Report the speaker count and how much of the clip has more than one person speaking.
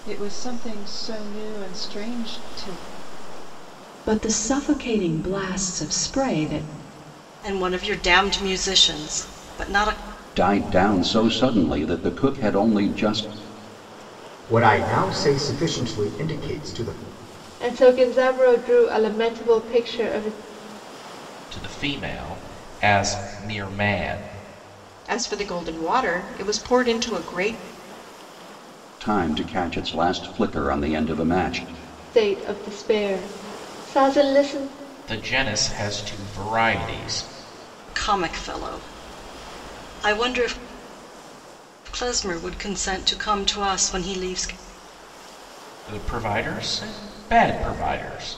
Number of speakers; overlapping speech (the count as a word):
eight, no overlap